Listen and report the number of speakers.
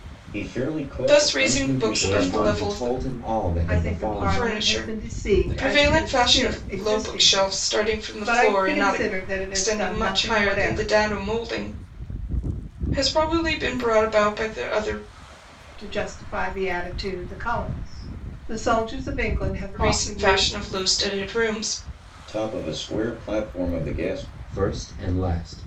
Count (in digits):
4